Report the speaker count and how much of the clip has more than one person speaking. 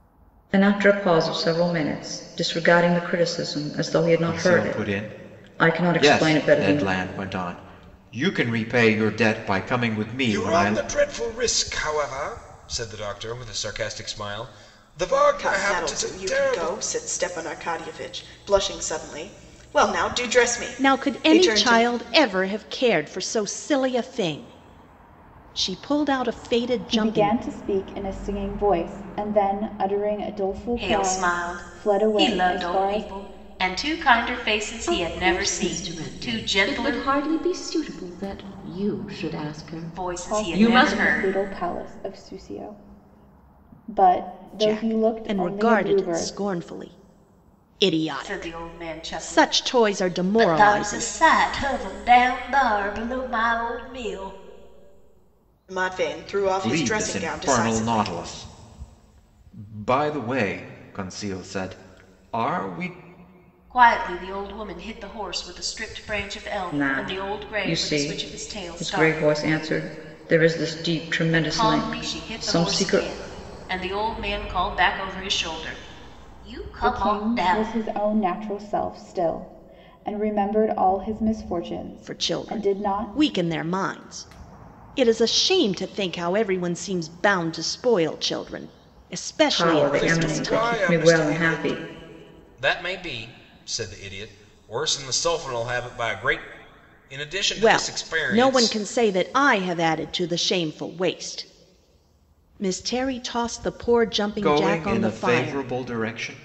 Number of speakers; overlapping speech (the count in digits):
8, about 29%